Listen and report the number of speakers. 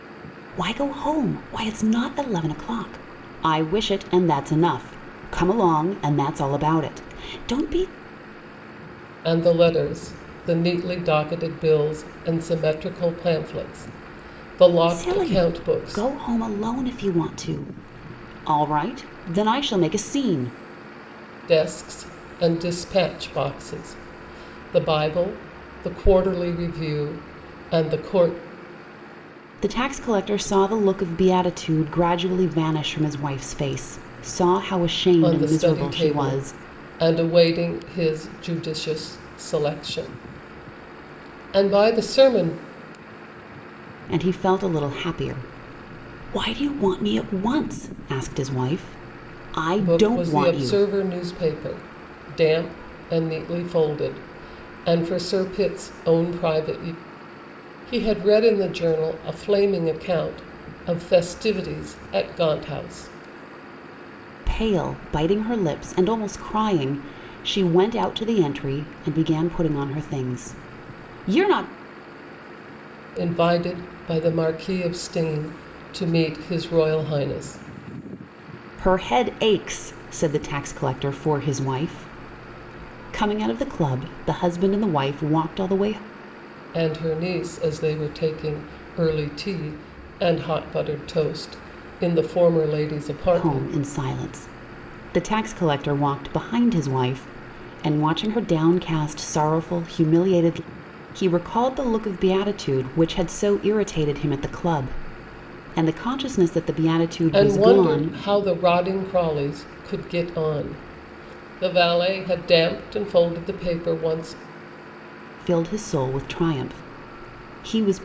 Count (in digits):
2